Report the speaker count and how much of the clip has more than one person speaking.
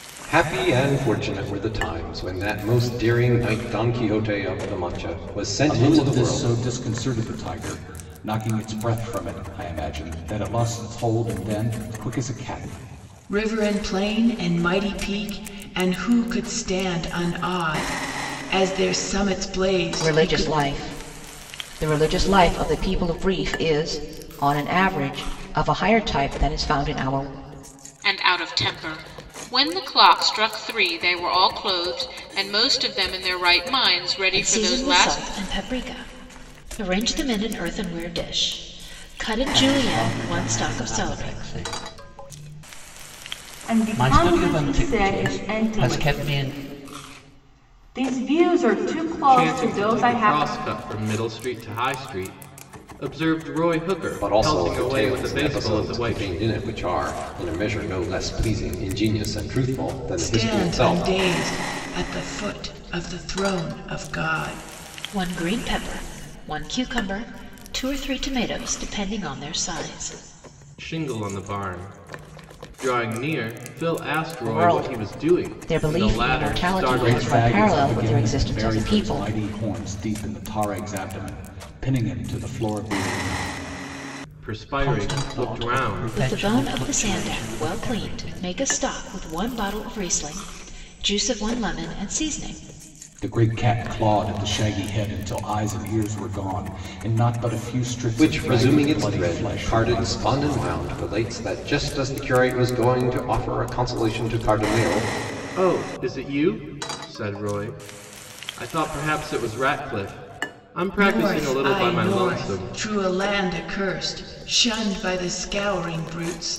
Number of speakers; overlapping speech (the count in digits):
9, about 21%